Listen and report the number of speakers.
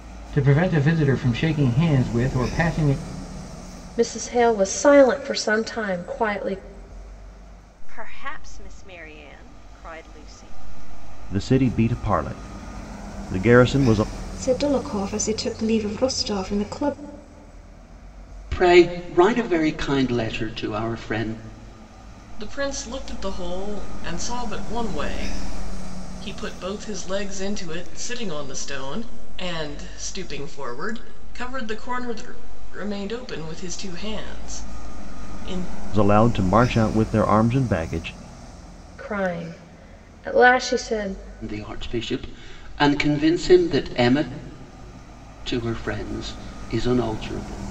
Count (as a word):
seven